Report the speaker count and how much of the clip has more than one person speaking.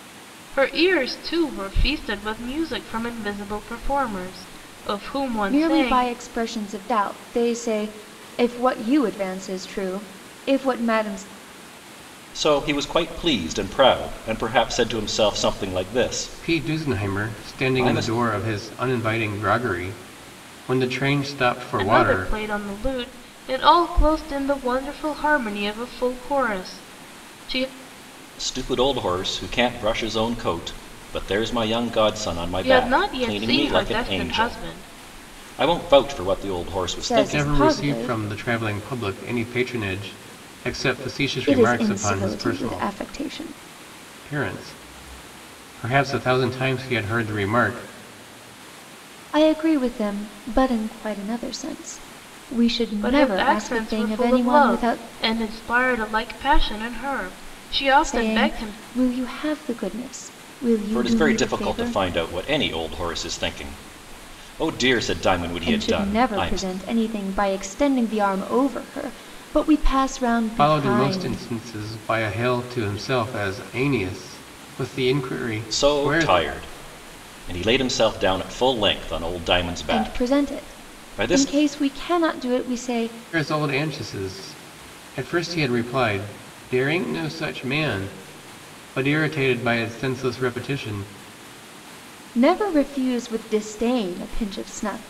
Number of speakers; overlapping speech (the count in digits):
4, about 17%